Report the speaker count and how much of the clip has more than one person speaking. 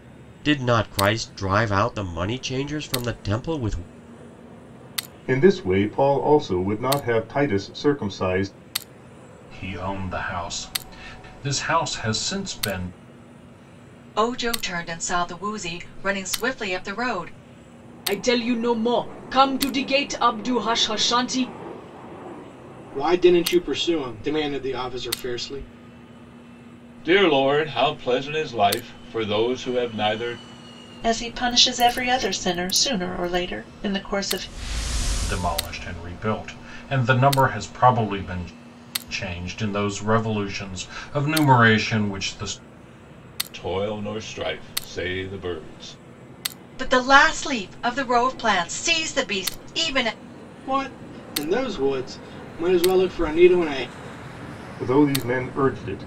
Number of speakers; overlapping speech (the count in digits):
8, no overlap